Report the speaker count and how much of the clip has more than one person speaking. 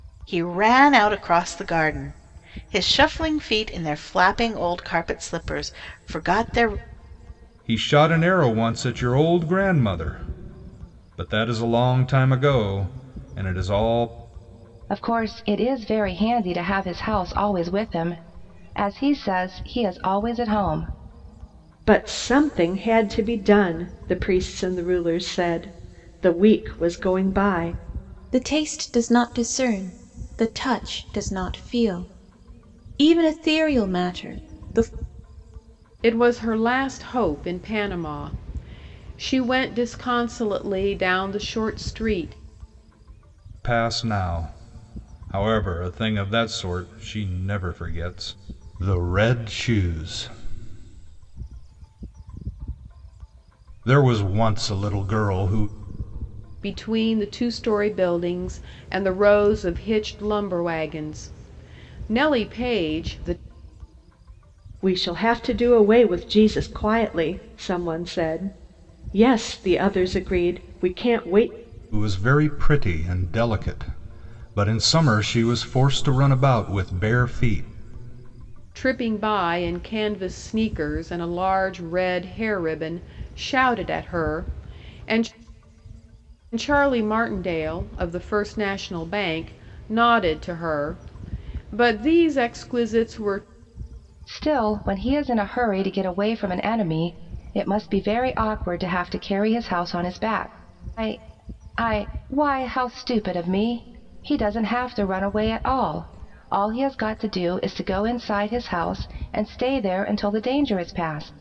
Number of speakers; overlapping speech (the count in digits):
6, no overlap